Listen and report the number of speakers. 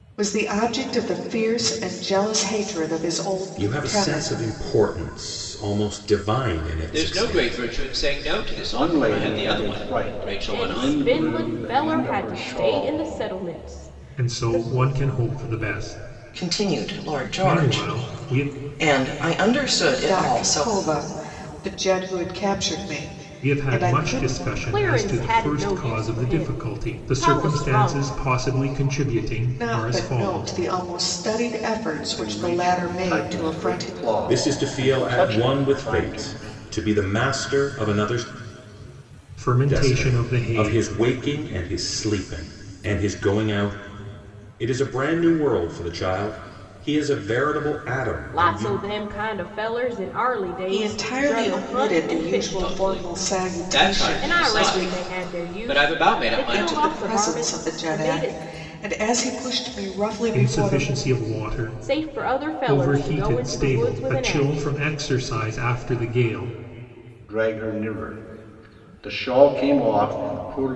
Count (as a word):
seven